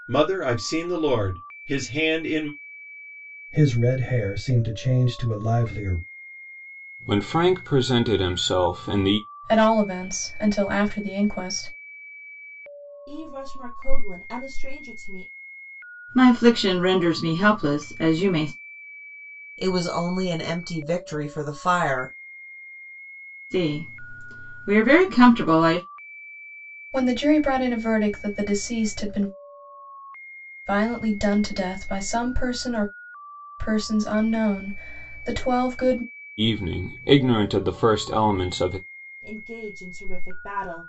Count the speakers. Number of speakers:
7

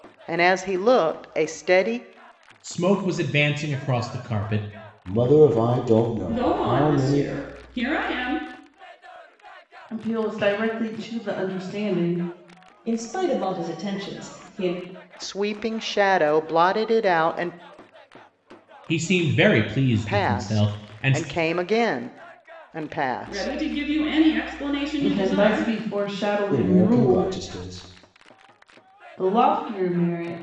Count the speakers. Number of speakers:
6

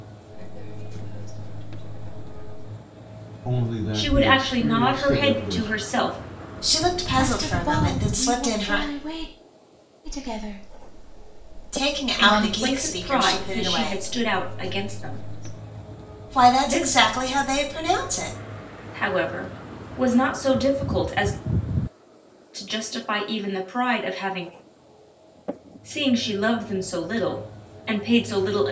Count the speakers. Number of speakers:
5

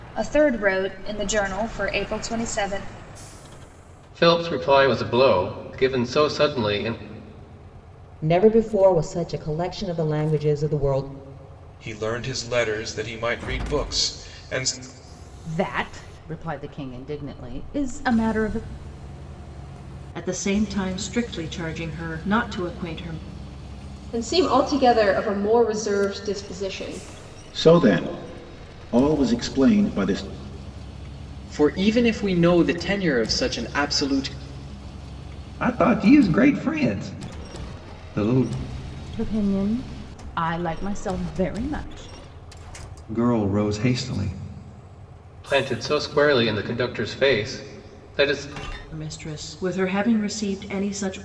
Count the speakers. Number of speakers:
10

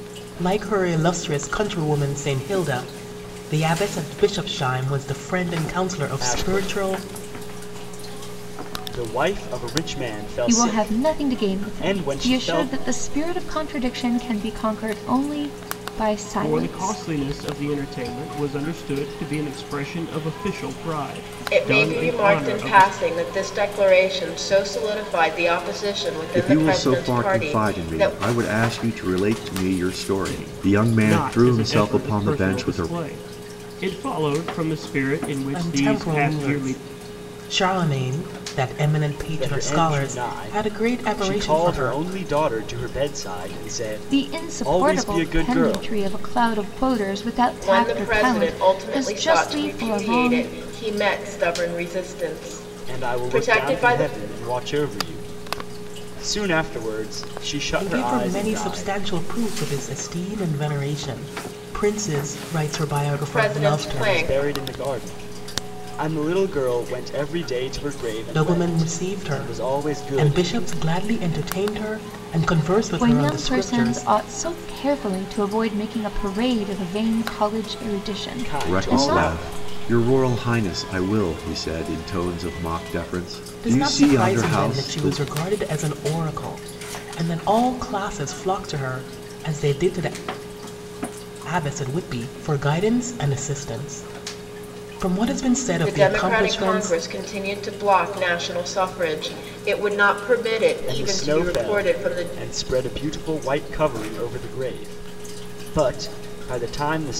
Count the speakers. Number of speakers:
6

